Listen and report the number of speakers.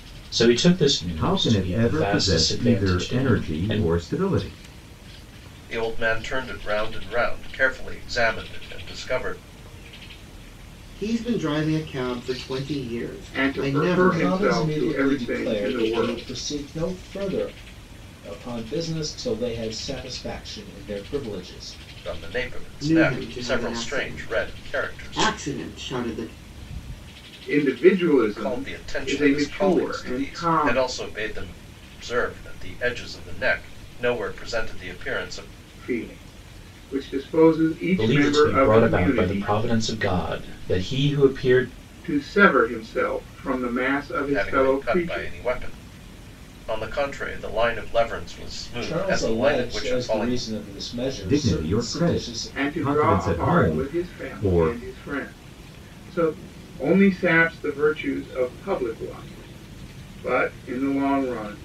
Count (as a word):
six